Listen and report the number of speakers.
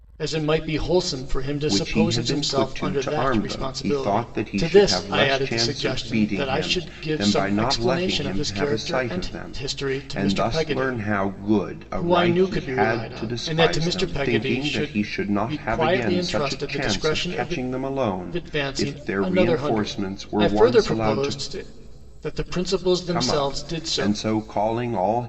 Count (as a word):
two